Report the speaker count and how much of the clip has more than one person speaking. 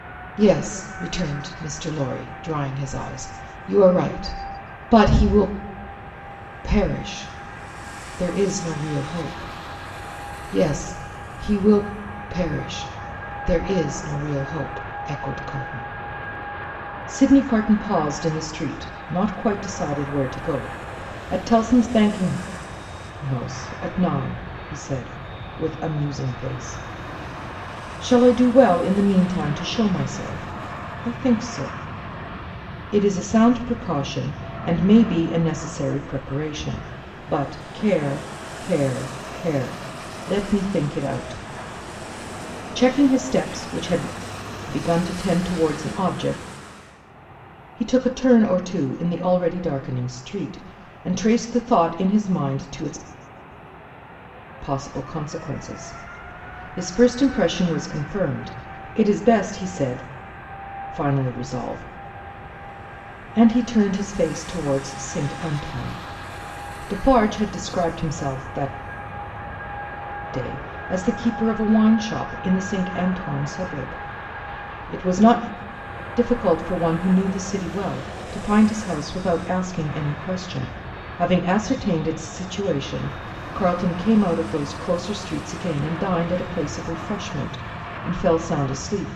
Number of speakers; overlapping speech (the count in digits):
1, no overlap